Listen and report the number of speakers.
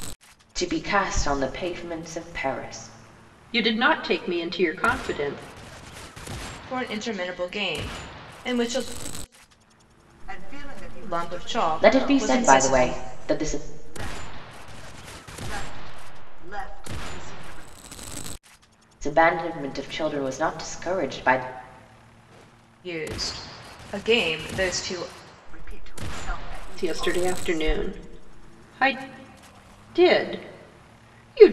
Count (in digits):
4